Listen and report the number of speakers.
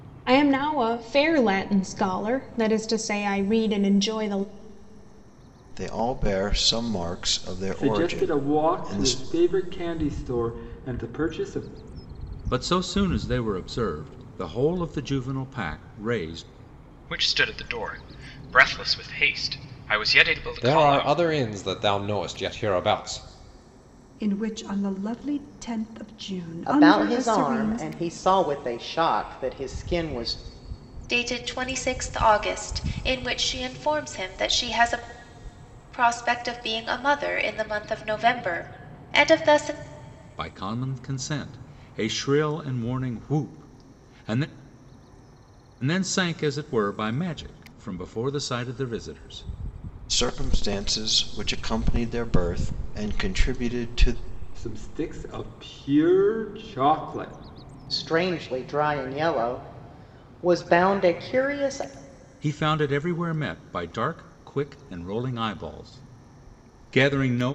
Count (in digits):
9